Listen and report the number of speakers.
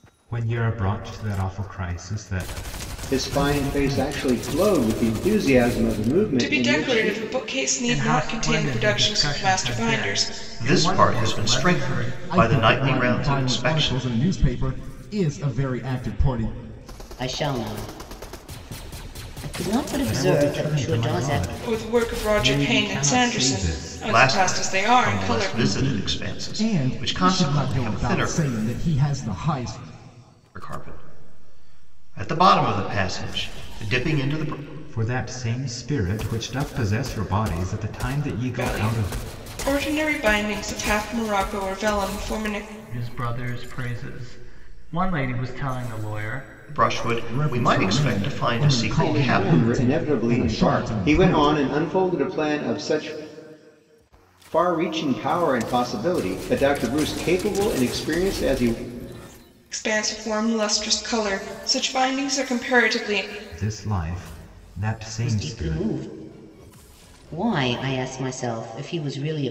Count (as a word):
seven